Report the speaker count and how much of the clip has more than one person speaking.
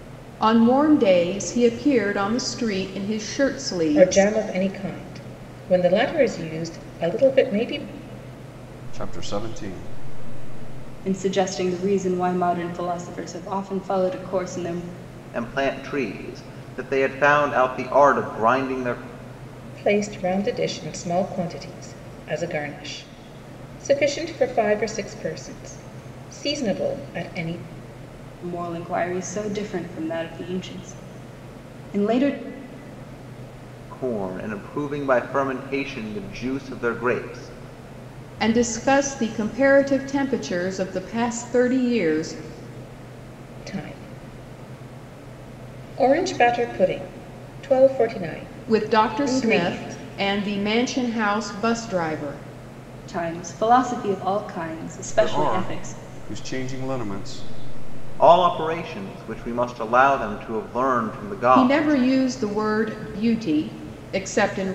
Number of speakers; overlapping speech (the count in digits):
5, about 5%